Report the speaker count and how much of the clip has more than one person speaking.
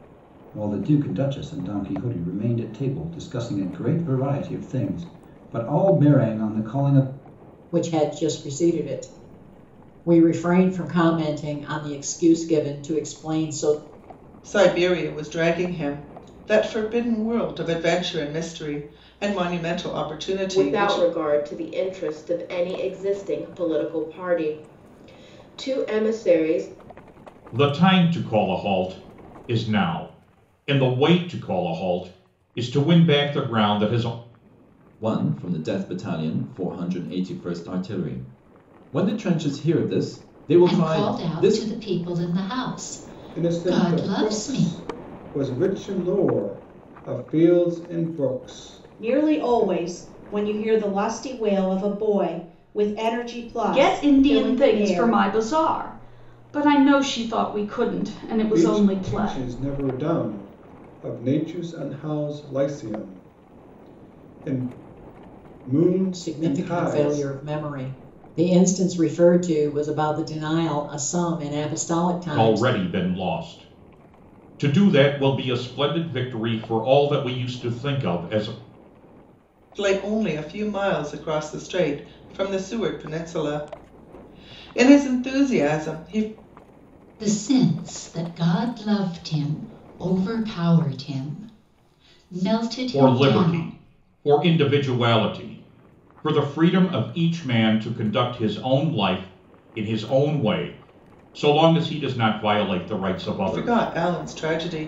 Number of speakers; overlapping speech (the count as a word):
ten, about 9%